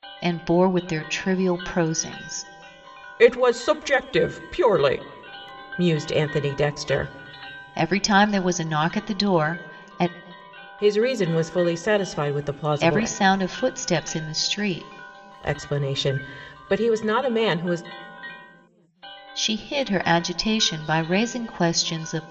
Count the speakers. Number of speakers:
two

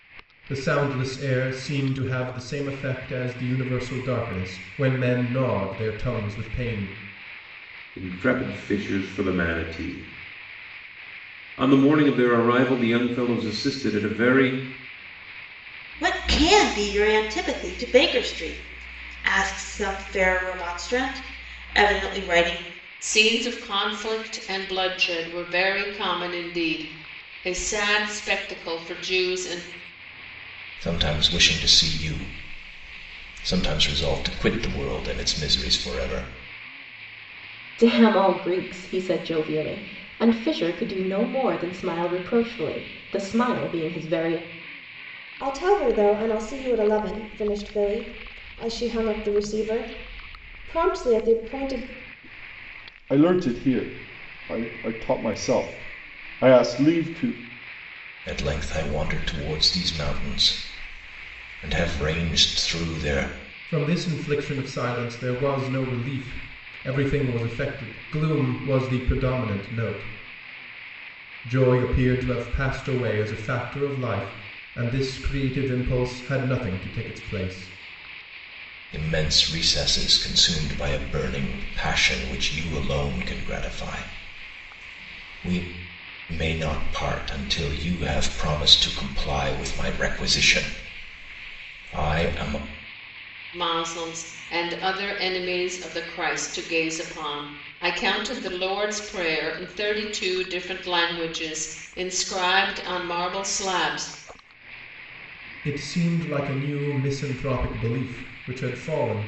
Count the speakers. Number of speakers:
eight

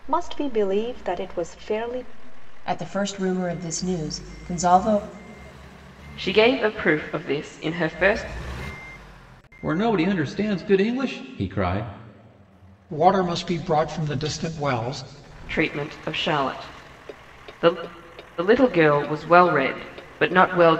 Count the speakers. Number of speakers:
five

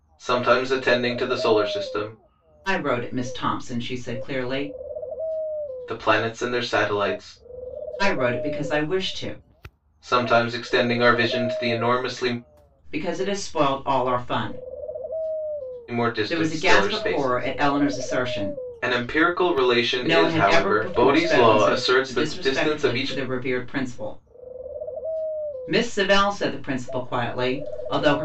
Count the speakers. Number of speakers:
two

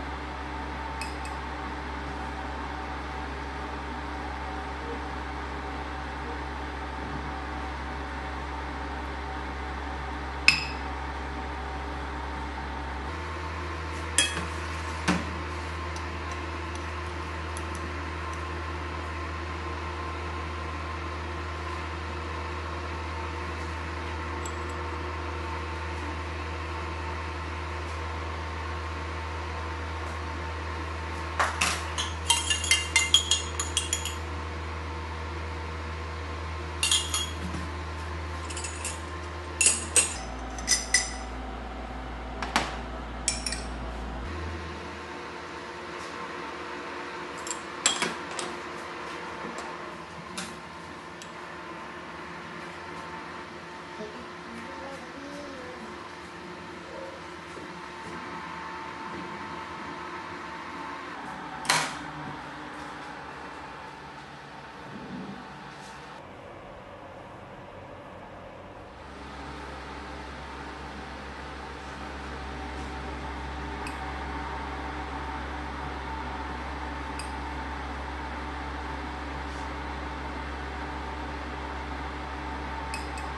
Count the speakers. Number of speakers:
zero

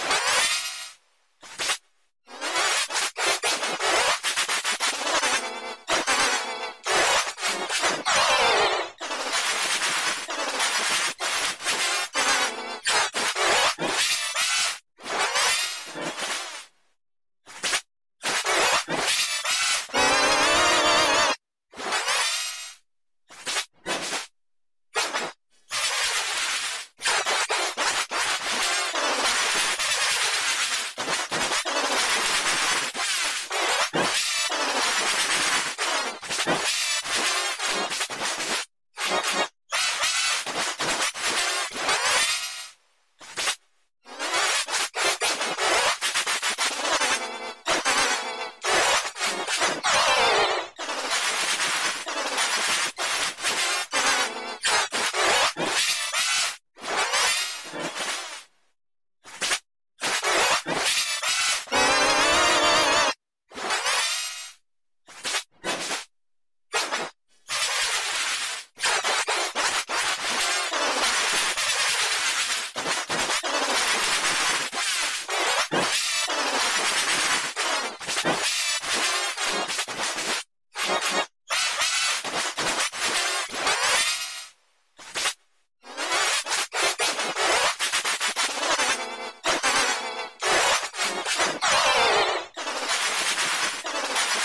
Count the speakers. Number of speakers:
zero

